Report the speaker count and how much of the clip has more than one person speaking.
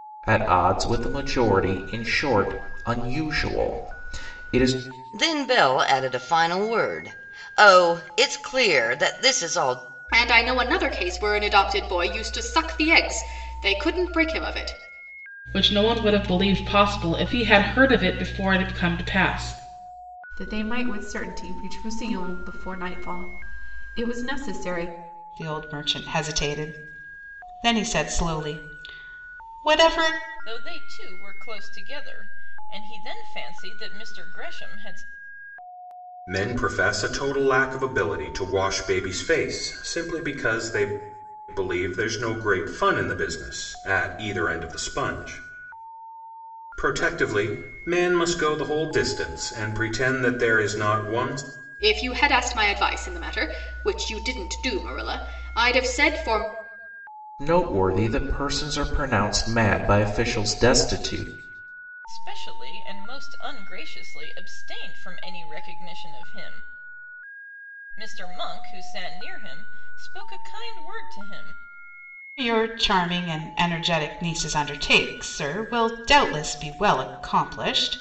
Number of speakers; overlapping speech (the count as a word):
eight, no overlap